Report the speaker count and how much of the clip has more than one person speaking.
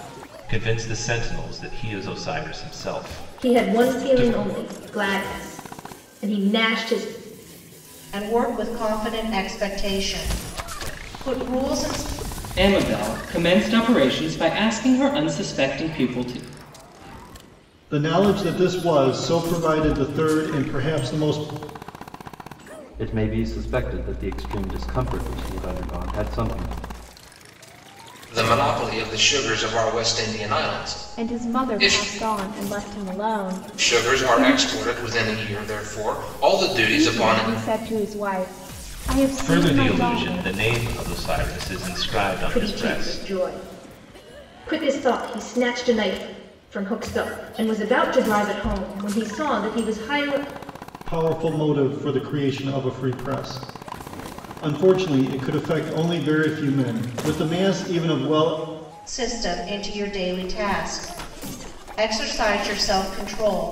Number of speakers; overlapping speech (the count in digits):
8, about 8%